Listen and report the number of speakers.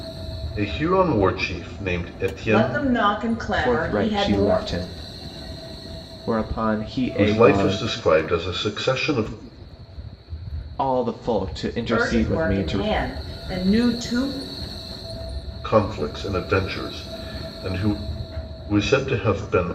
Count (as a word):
three